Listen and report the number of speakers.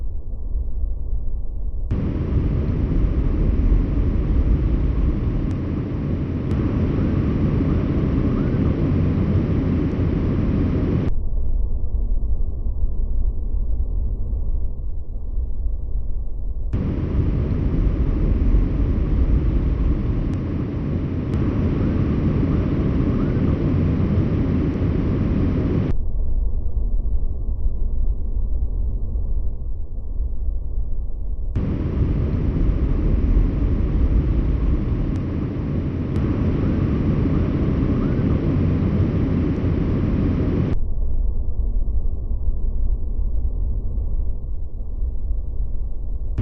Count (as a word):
zero